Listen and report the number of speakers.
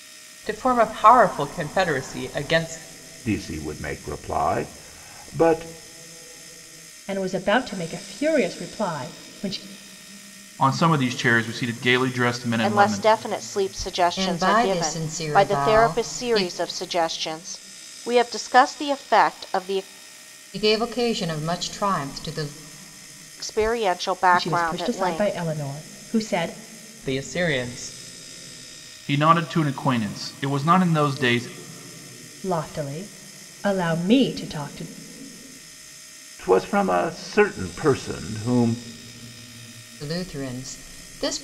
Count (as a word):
six